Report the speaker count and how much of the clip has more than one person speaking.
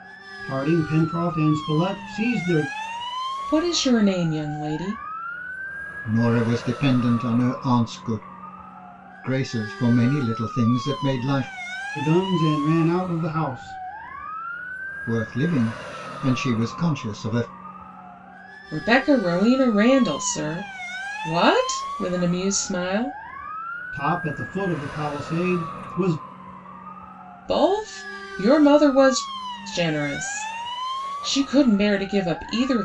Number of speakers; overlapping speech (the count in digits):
3, no overlap